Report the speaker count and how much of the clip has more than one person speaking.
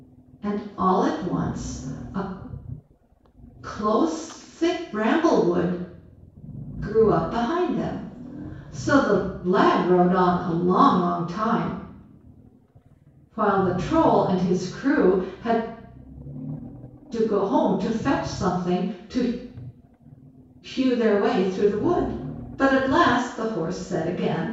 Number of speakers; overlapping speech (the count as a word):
one, no overlap